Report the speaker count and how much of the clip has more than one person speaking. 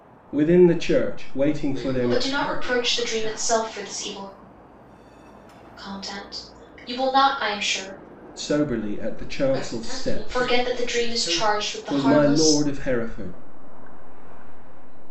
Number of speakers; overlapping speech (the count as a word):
four, about 49%